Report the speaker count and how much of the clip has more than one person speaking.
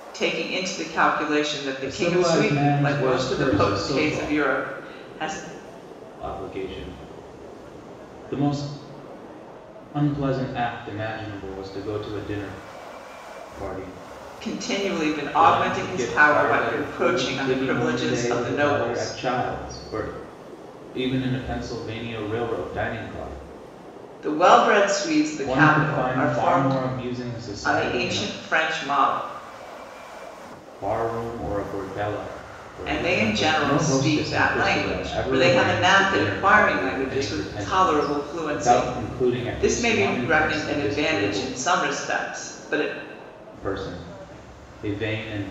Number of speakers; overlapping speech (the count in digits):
2, about 39%